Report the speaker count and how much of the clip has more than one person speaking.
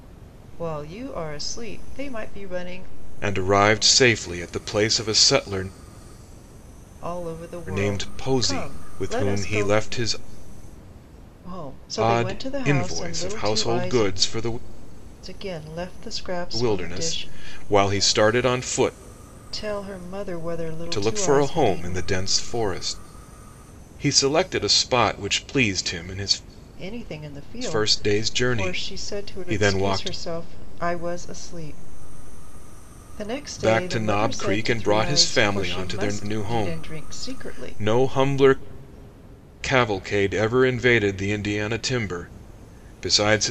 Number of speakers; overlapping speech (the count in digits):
2, about 30%